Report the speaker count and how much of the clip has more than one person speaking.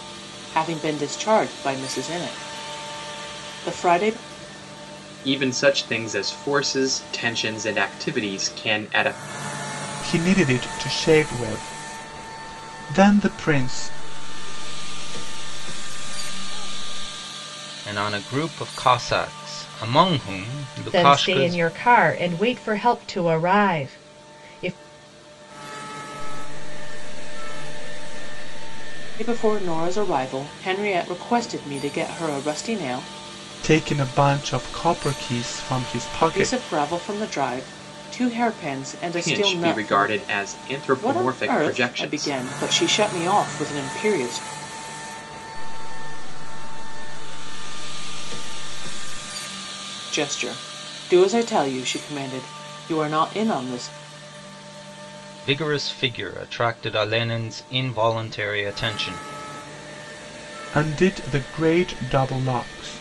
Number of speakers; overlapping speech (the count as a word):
six, about 8%